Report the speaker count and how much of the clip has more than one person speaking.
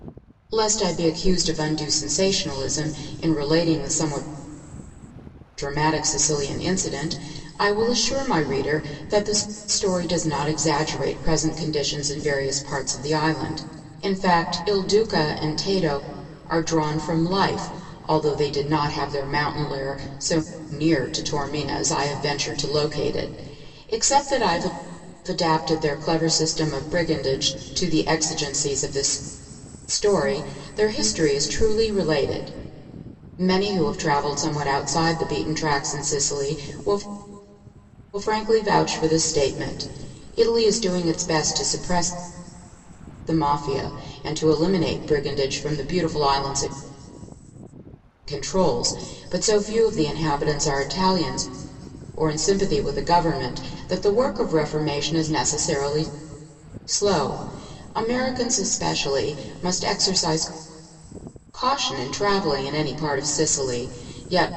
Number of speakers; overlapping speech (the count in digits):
1, no overlap